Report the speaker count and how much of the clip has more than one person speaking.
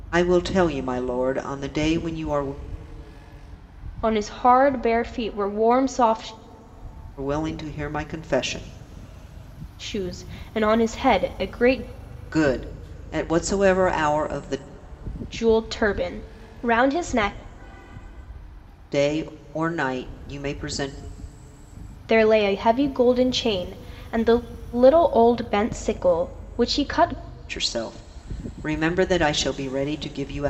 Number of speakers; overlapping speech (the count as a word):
two, no overlap